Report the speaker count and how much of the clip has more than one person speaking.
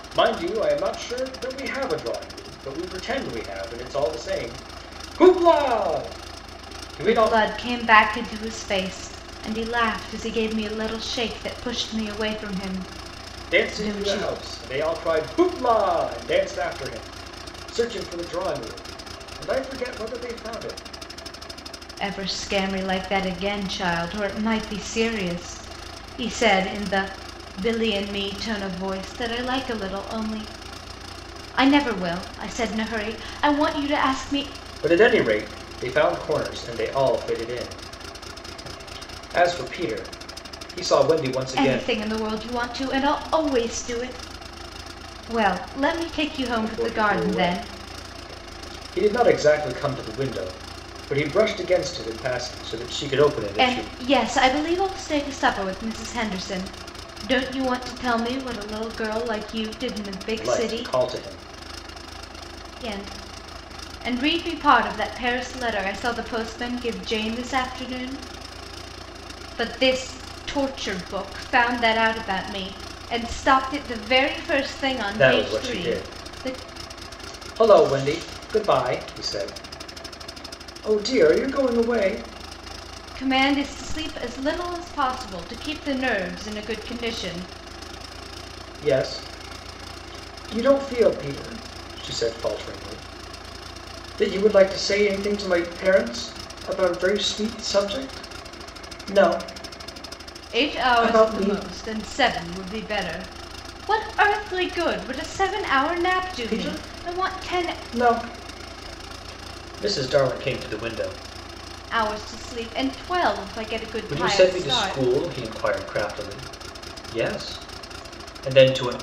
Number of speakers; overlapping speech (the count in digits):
2, about 7%